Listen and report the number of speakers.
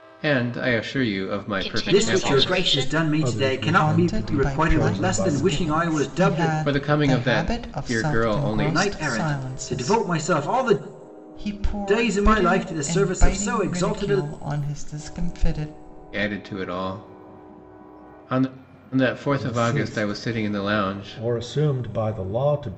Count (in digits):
5